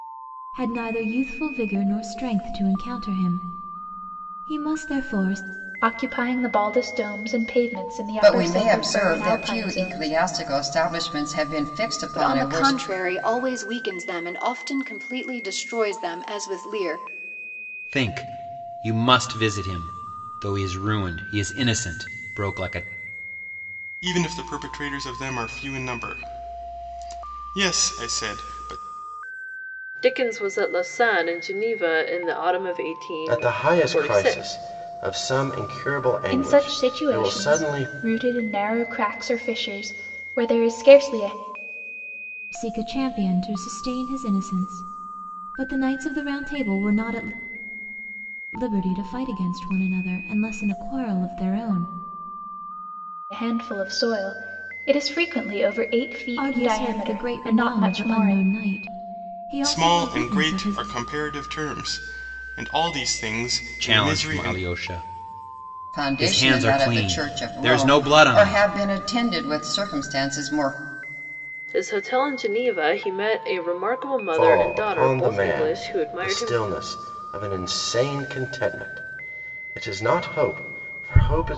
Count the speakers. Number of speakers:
8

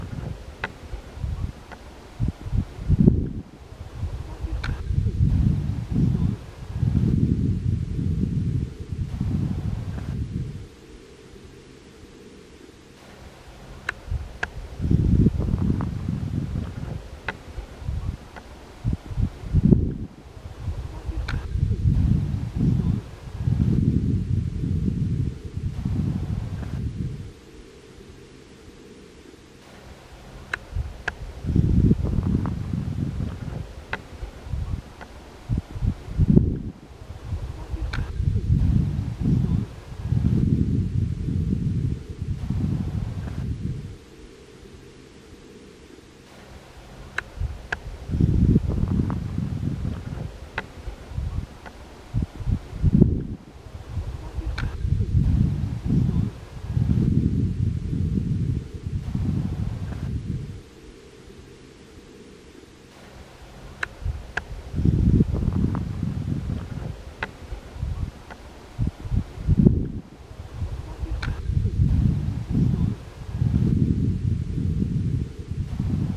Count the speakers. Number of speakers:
0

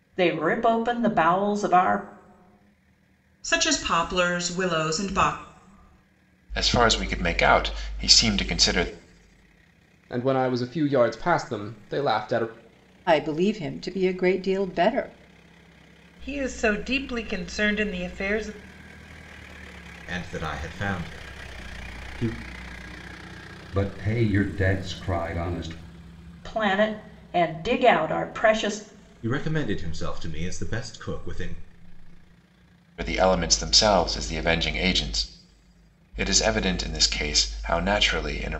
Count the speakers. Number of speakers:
8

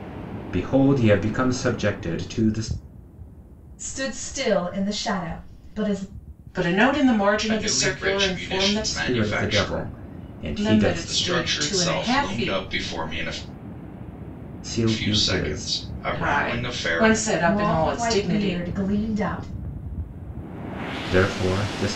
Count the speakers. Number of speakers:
4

